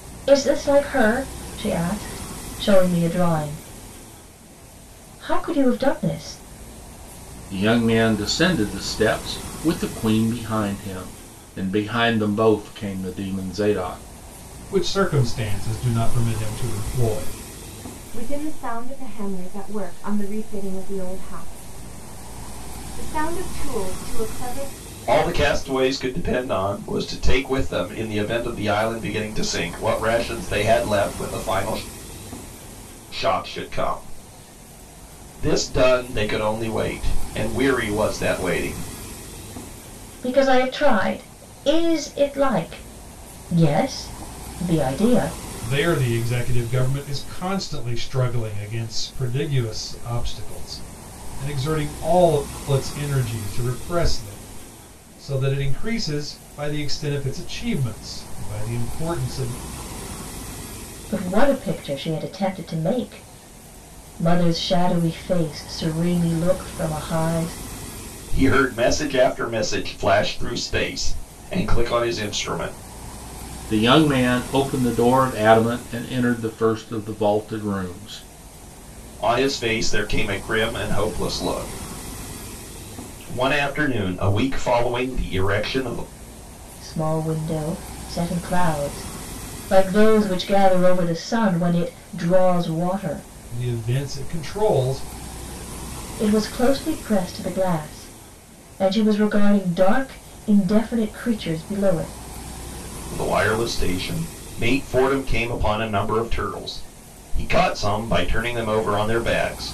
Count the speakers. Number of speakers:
5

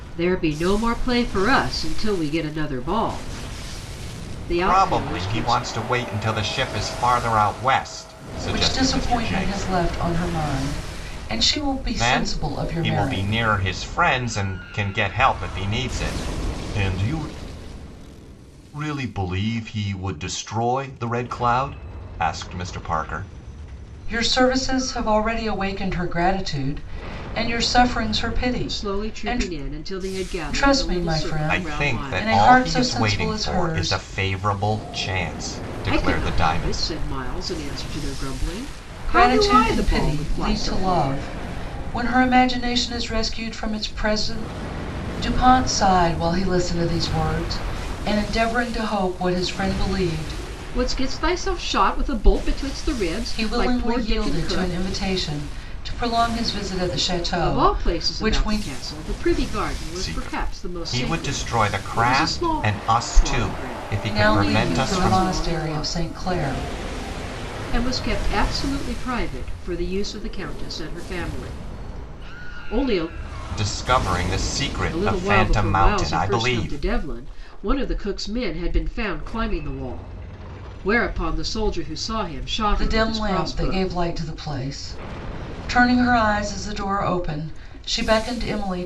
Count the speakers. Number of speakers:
3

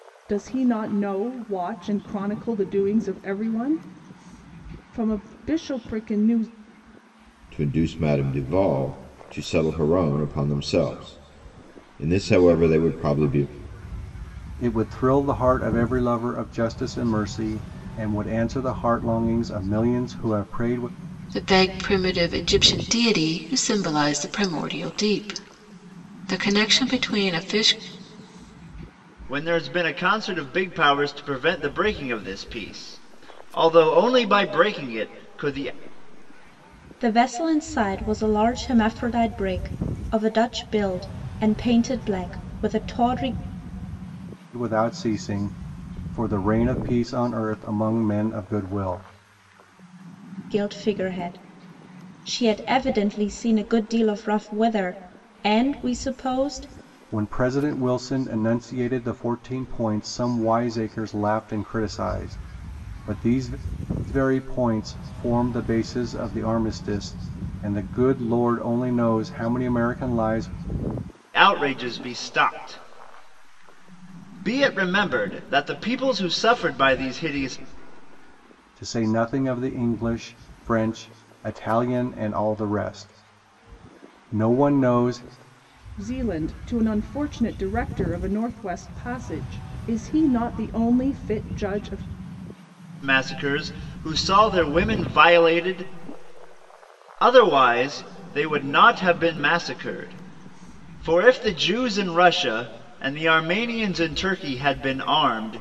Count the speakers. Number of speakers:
6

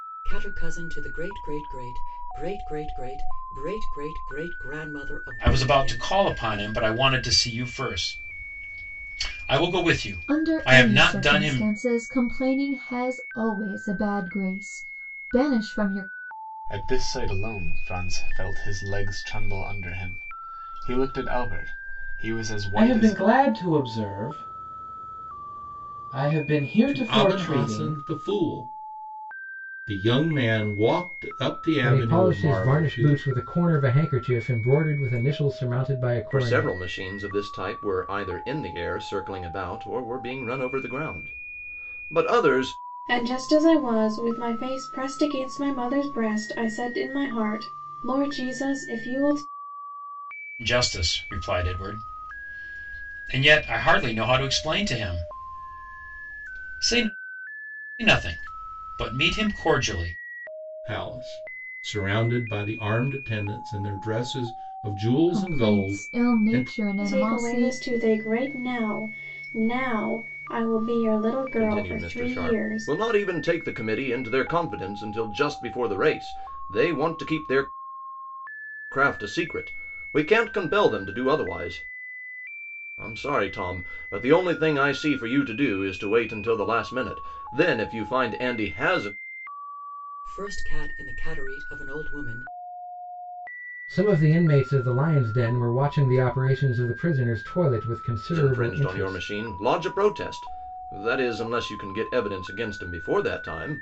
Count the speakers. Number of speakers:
9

